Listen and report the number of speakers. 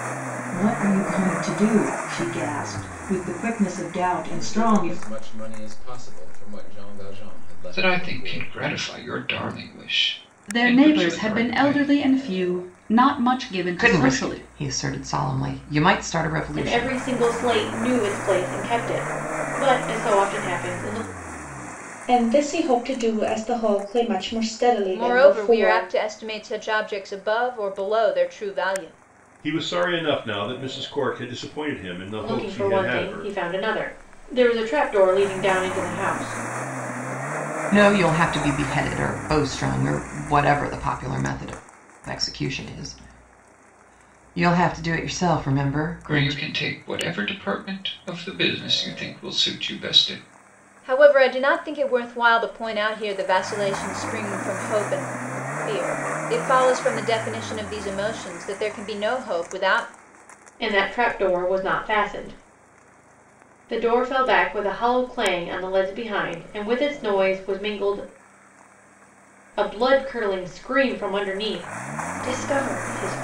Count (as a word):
nine